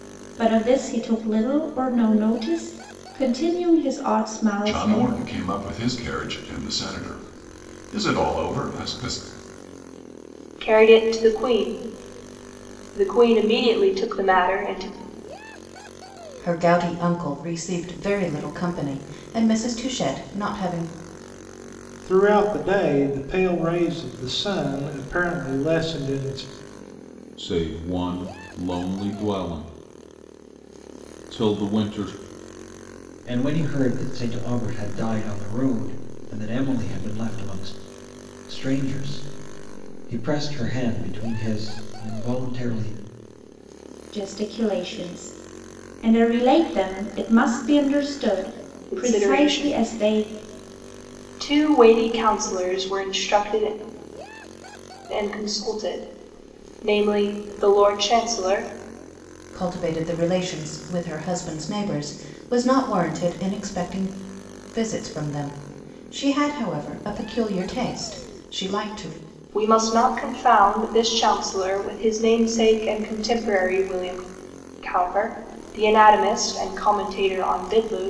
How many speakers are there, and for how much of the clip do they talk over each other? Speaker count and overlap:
seven, about 2%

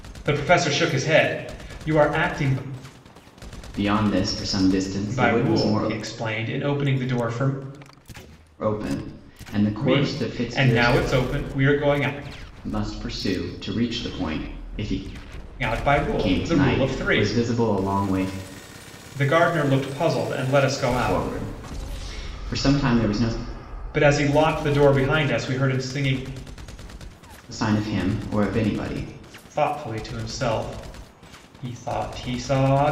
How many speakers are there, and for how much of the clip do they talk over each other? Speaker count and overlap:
two, about 11%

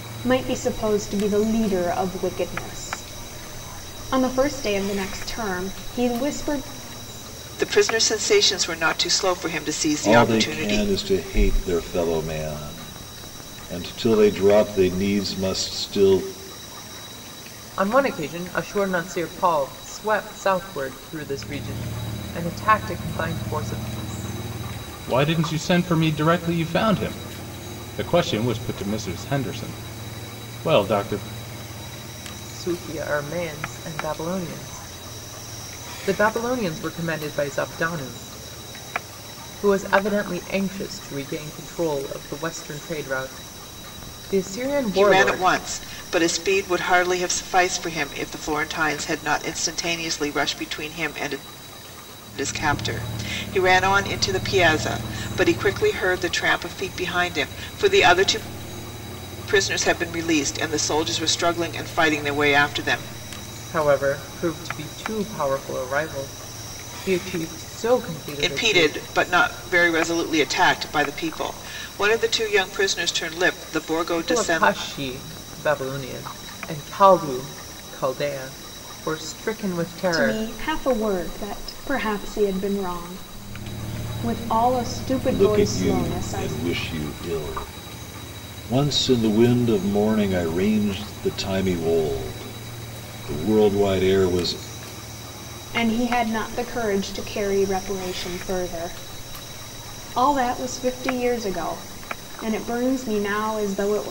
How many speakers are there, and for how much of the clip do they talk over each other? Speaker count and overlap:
five, about 4%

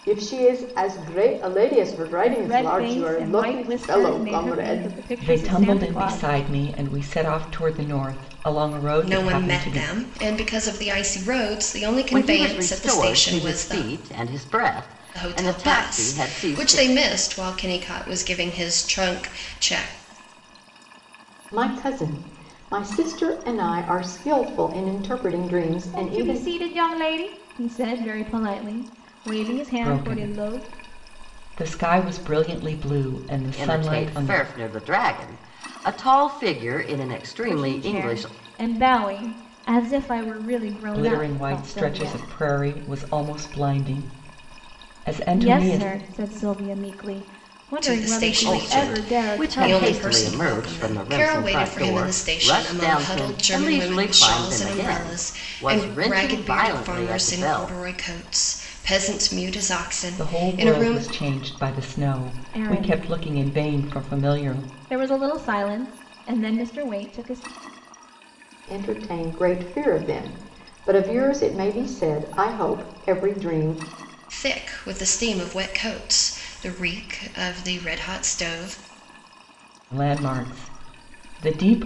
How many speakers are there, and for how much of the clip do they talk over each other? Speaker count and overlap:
five, about 32%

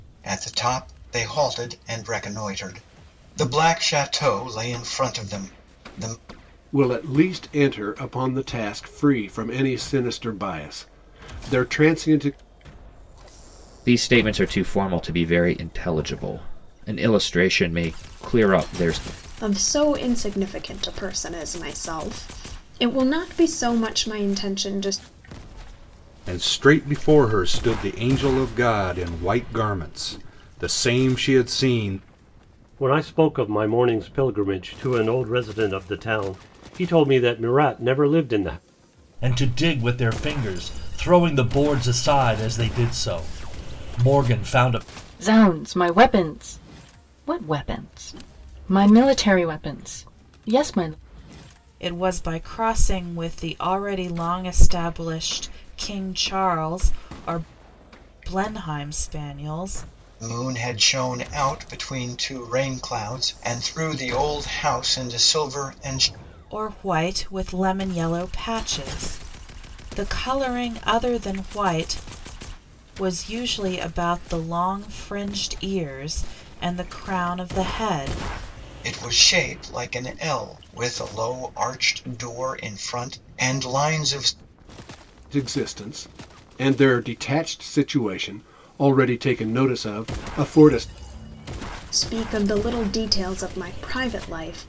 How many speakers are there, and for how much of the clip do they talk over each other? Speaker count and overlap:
nine, no overlap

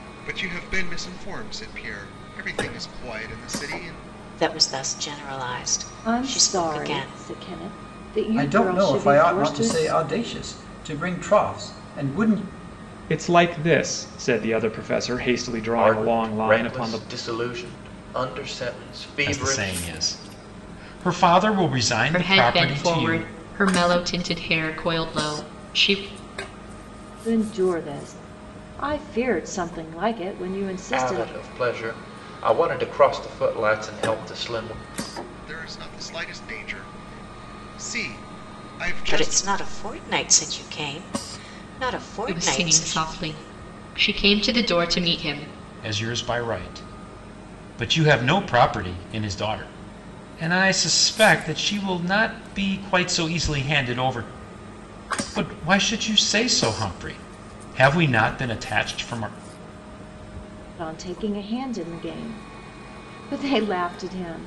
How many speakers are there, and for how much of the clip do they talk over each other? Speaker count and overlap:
eight, about 11%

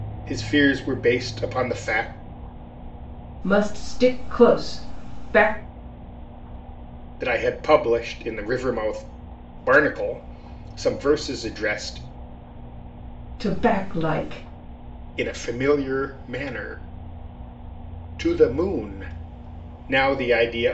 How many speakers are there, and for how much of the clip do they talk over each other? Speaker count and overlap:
two, no overlap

